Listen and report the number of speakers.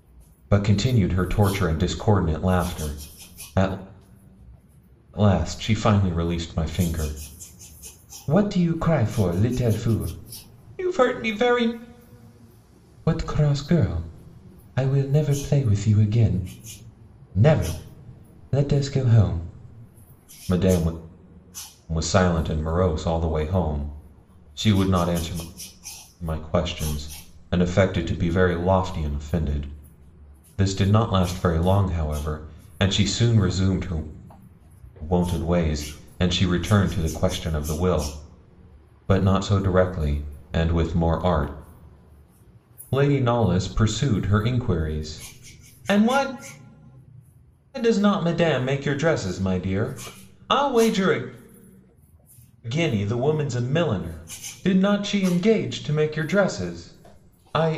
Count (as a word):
one